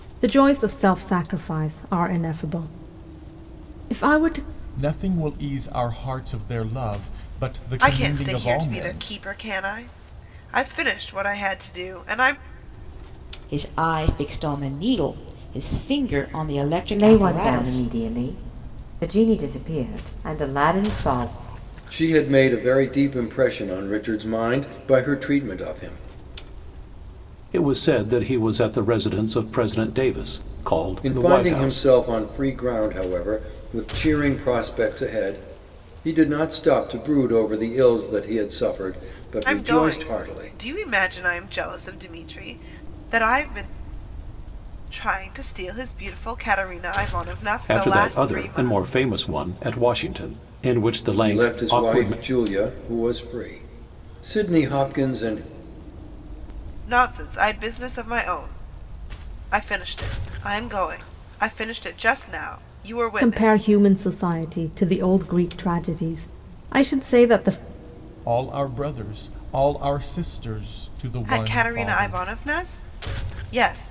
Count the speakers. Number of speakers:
7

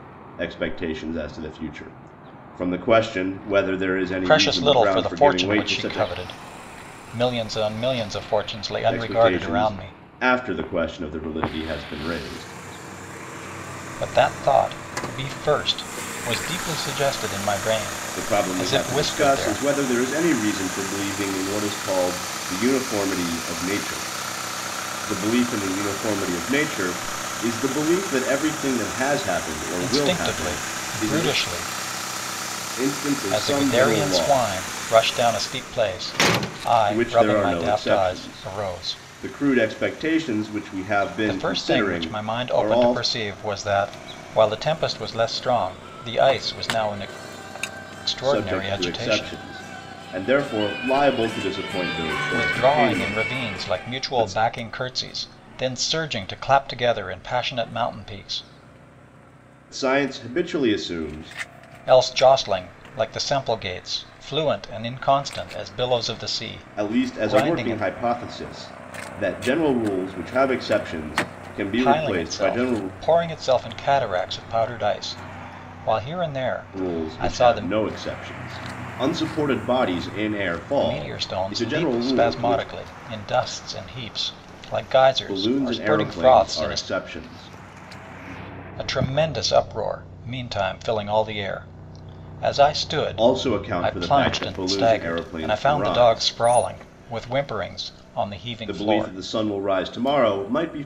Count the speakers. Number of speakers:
2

